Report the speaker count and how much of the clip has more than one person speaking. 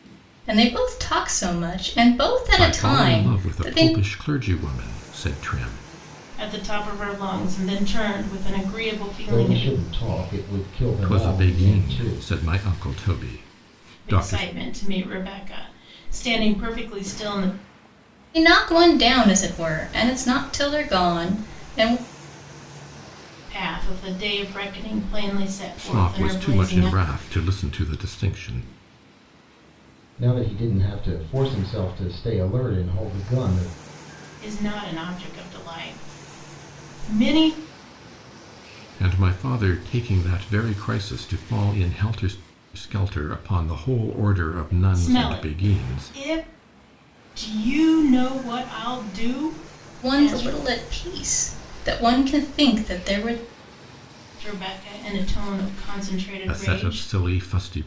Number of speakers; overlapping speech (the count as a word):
four, about 12%